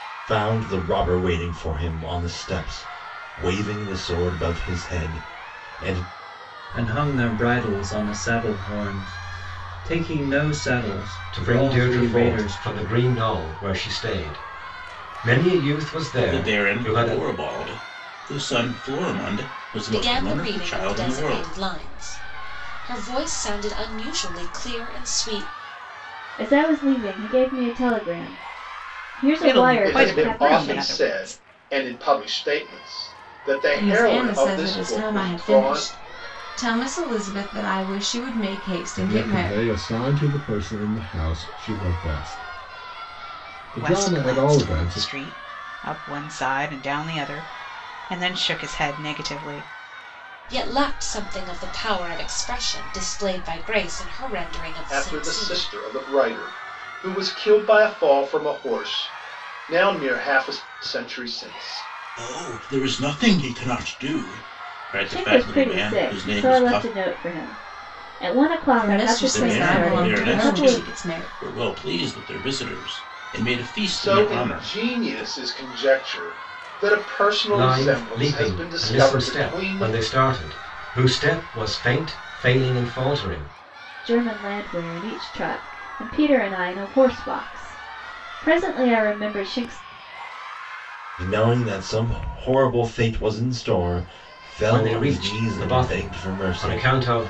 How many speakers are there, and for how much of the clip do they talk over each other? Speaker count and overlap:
ten, about 23%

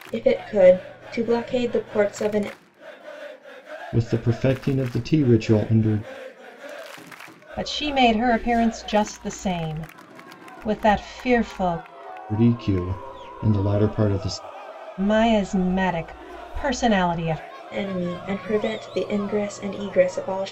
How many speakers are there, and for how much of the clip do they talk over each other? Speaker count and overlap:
three, no overlap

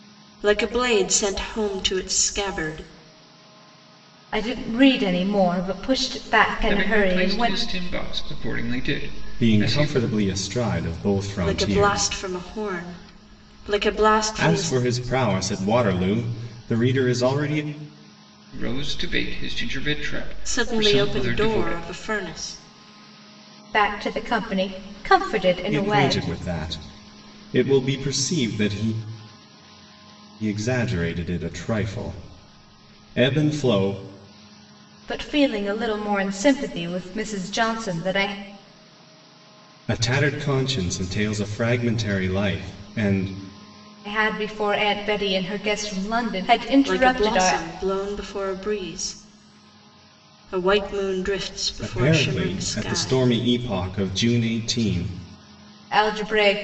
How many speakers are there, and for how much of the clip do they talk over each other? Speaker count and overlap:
four, about 12%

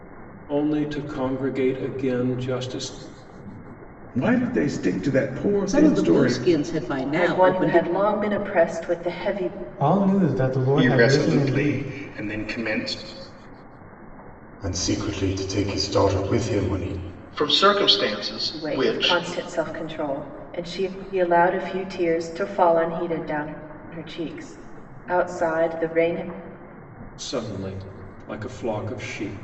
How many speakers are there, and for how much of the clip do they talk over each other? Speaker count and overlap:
eight, about 11%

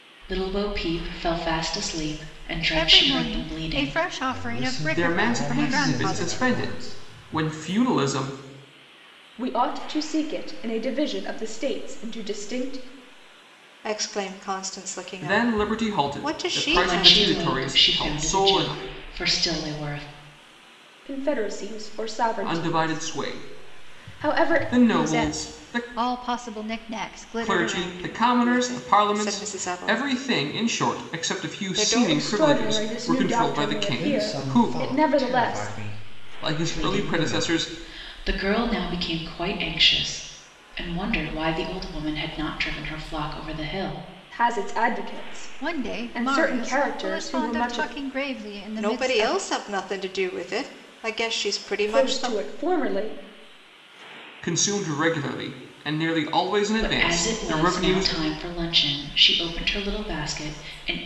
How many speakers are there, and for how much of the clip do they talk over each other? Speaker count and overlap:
six, about 42%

